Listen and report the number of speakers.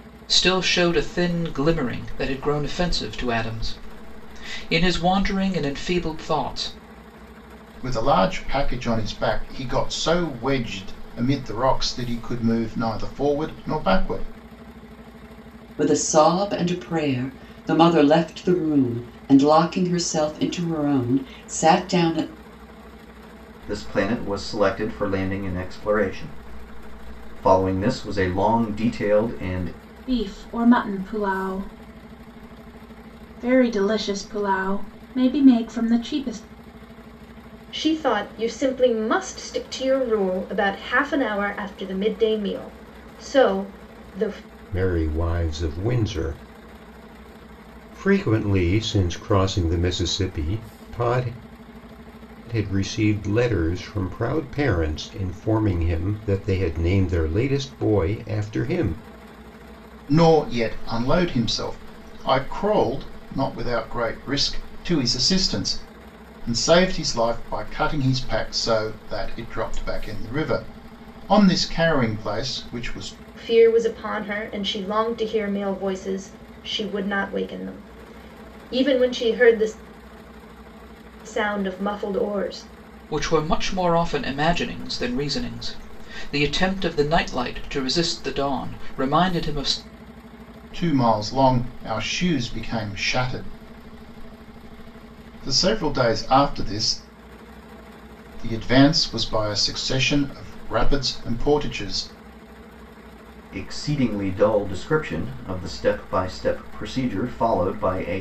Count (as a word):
seven